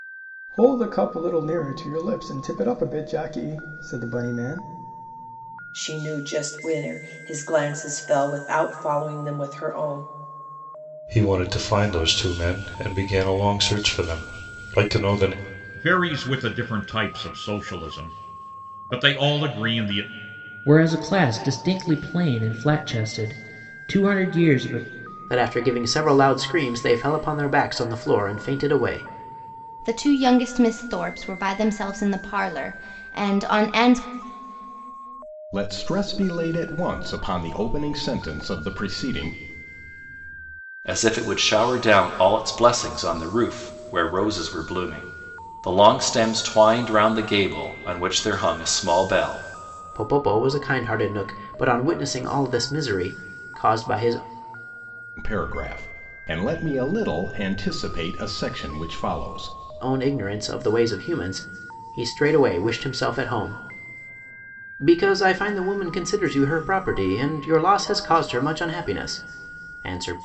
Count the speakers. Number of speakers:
nine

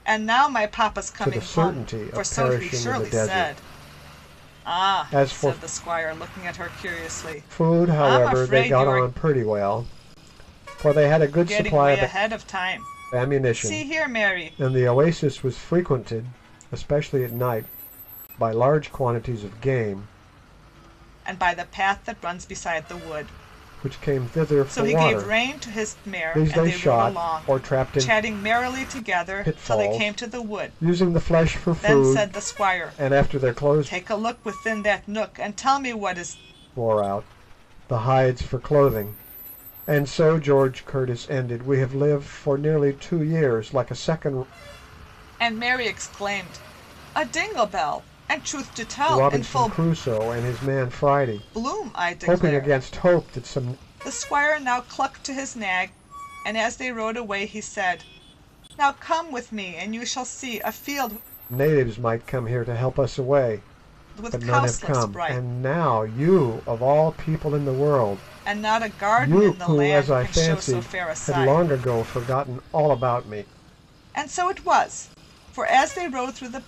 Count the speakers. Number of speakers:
two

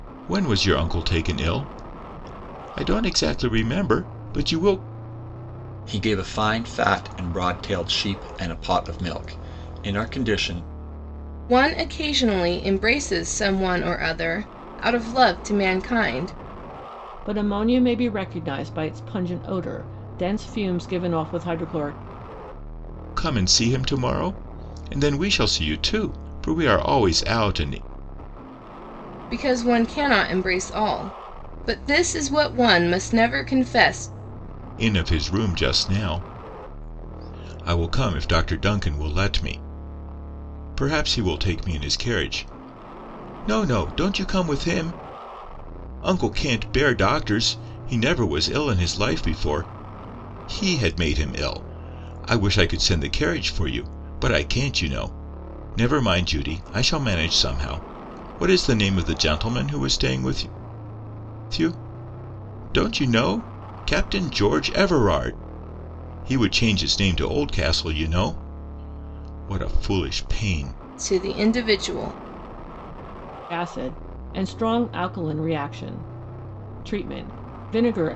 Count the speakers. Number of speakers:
four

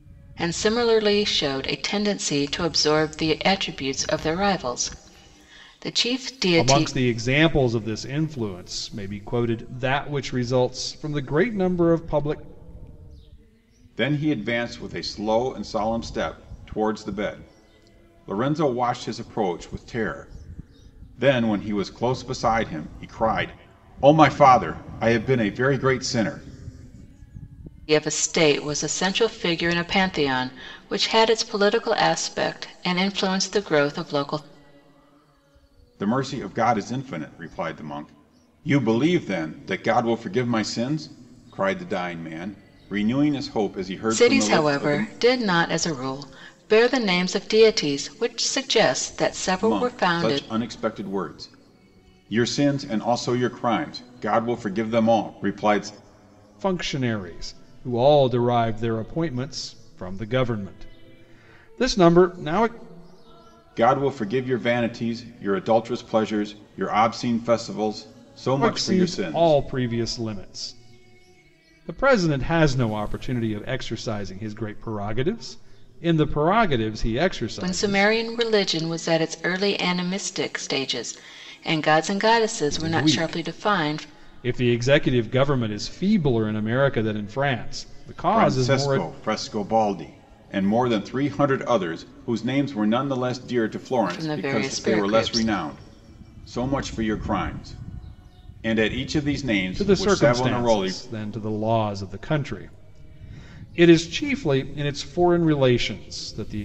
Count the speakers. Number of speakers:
three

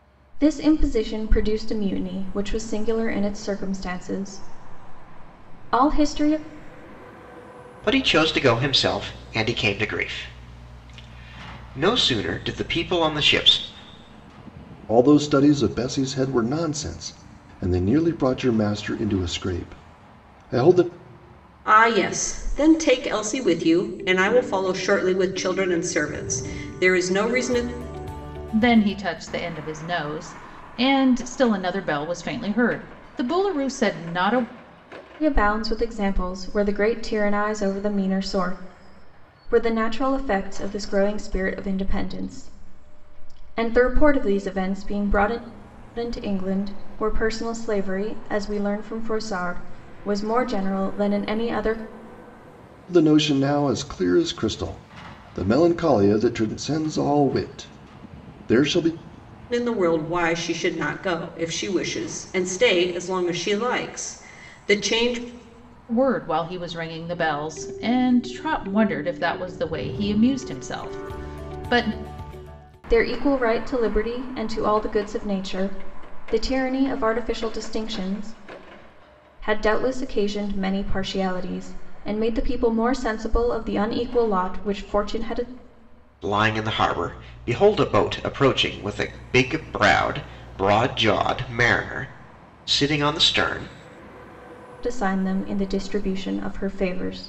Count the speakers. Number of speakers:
five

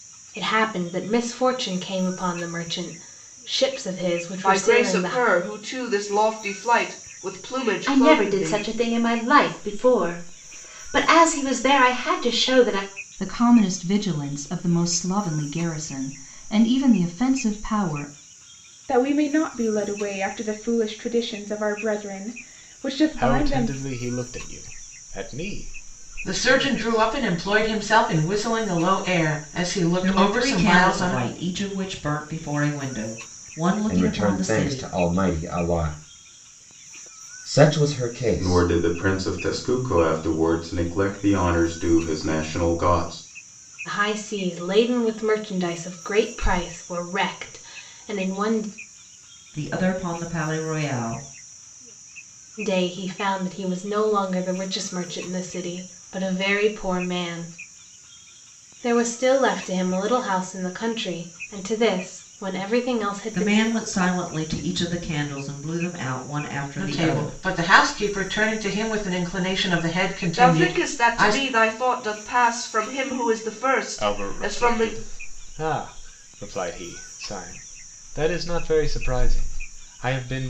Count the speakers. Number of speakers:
ten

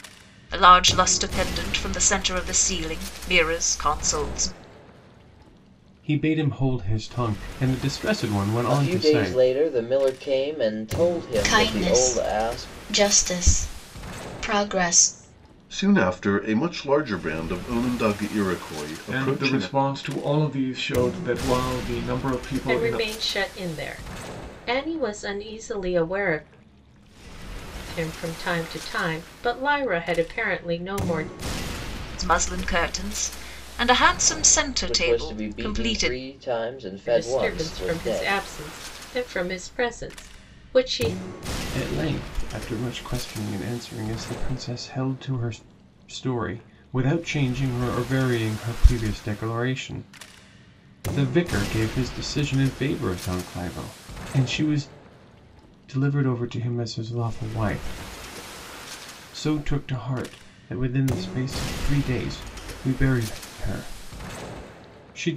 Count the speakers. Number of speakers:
seven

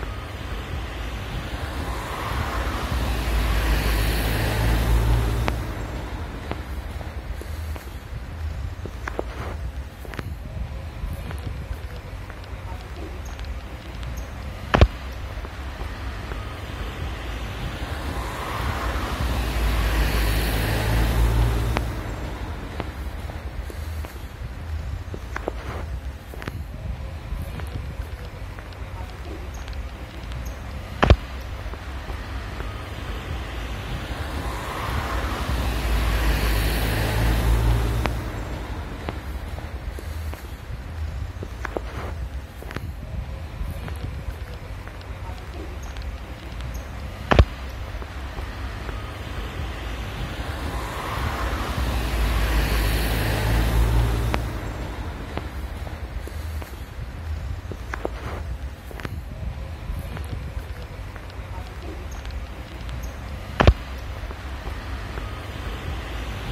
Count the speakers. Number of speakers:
zero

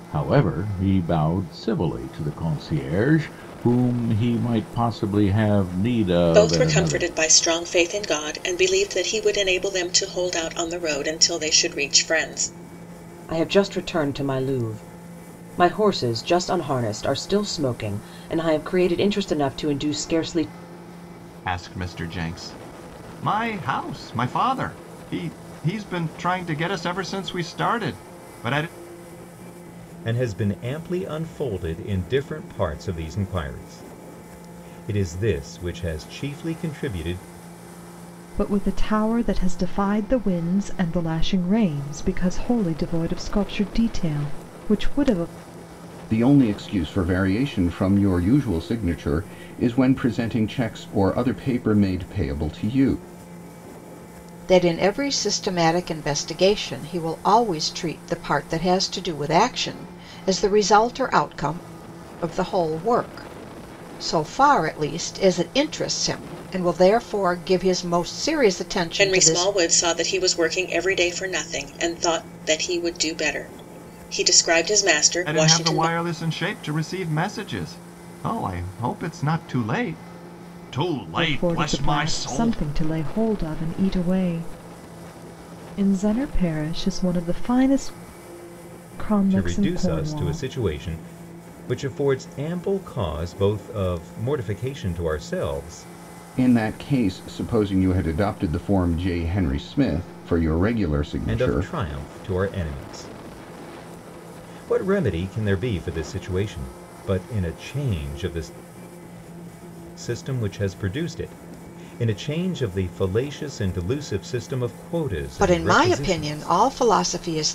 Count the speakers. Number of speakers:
eight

